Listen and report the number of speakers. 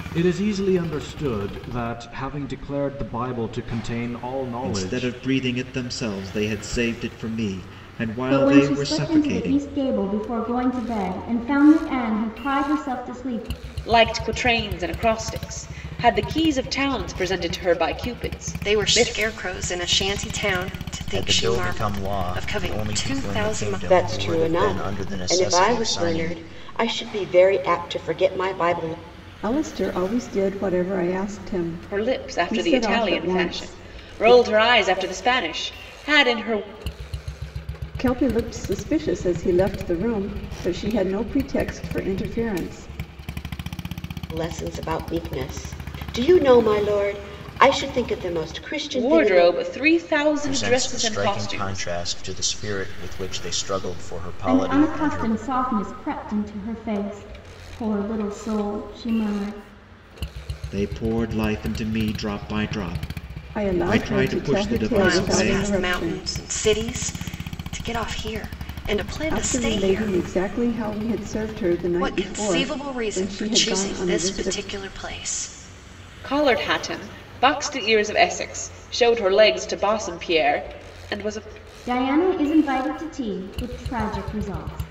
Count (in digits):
8